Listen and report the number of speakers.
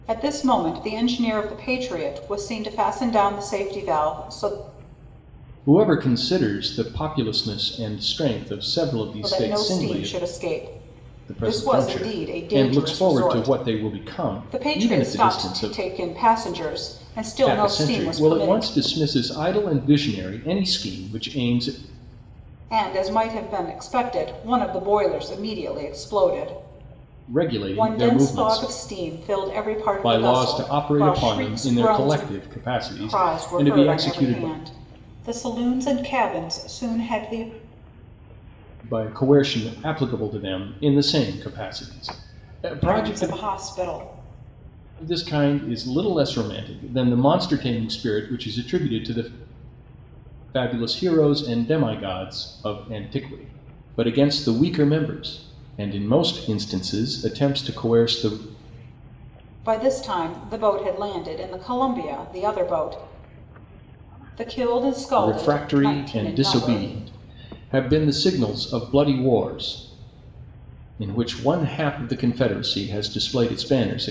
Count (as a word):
two